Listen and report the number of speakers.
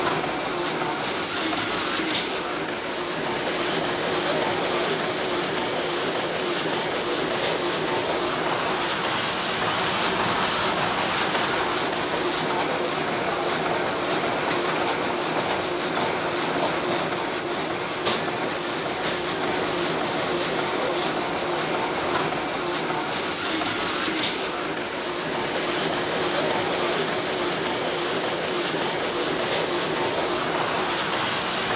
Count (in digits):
0